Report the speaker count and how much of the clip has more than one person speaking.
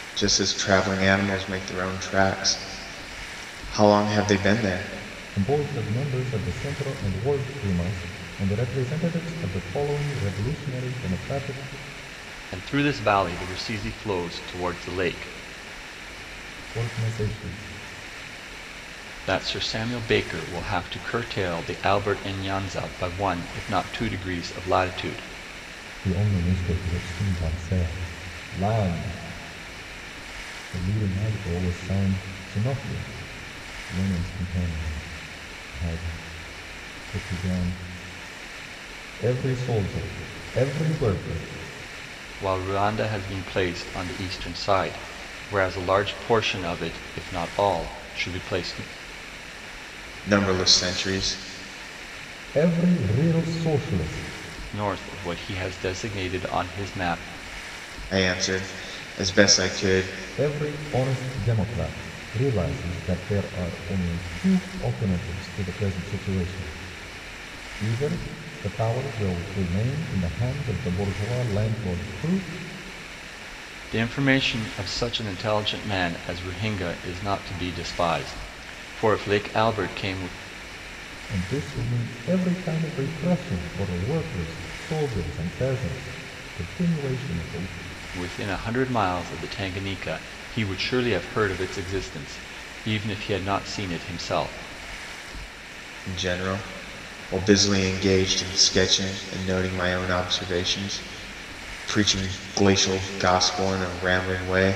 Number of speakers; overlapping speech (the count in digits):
3, no overlap